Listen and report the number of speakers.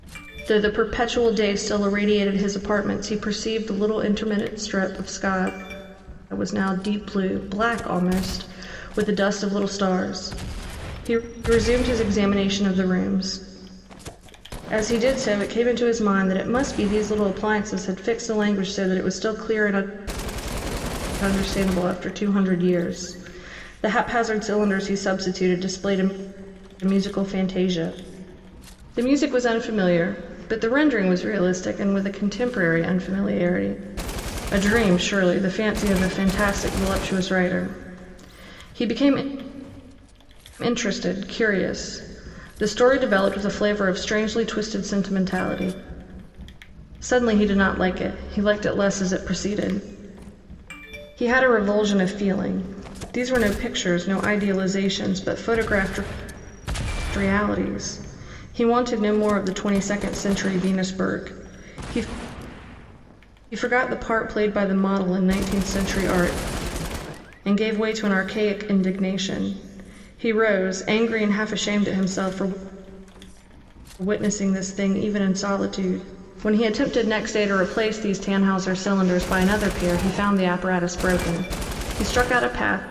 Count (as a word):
one